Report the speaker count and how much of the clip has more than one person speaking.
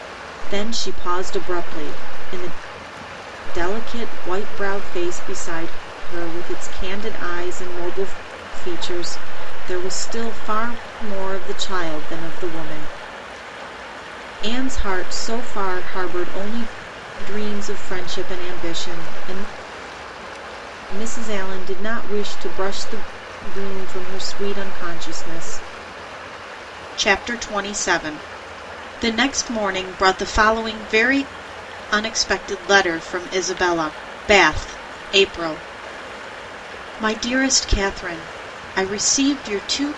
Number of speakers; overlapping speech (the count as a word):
one, no overlap